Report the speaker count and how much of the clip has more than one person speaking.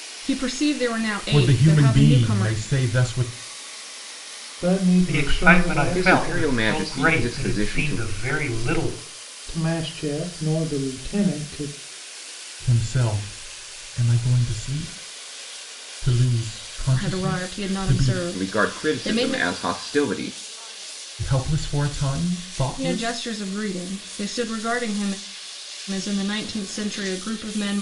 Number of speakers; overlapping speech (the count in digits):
5, about 25%